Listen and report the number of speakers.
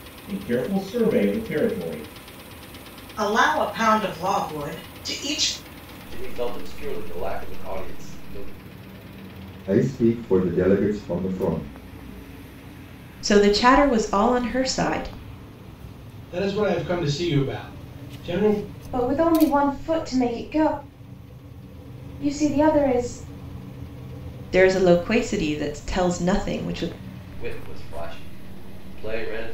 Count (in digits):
7